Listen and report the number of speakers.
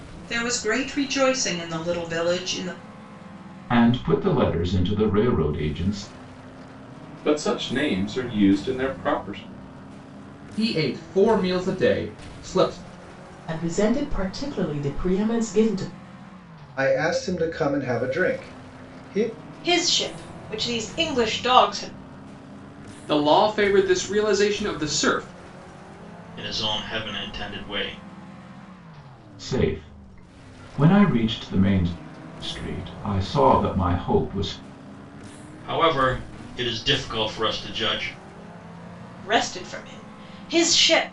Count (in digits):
9